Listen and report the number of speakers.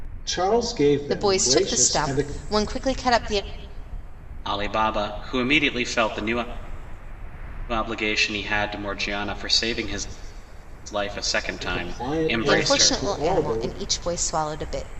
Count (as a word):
three